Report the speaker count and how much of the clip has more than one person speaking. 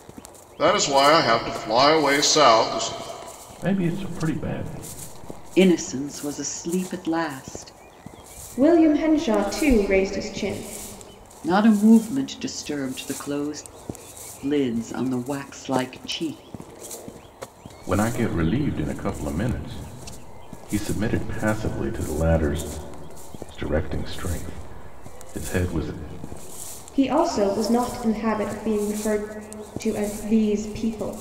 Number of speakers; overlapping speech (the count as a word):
four, no overlap